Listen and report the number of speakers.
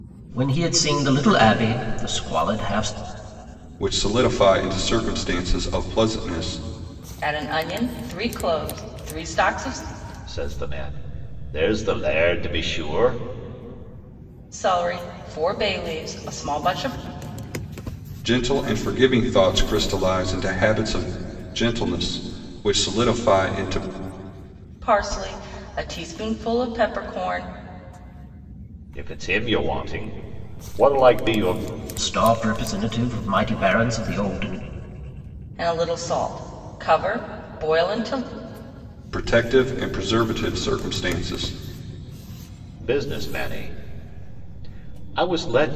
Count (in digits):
4